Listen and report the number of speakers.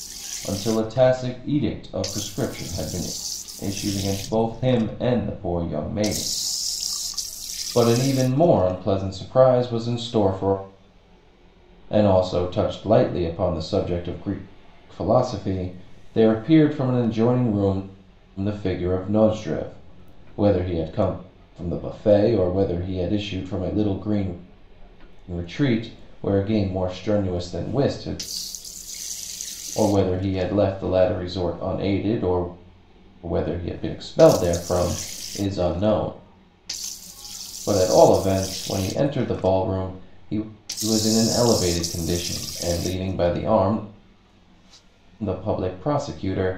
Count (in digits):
1